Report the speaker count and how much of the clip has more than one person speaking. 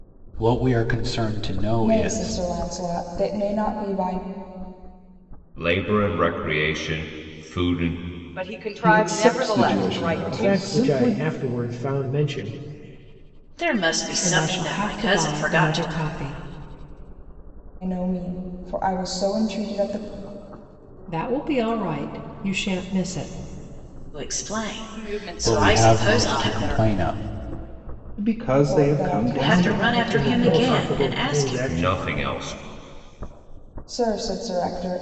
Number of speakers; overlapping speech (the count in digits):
8, about 29%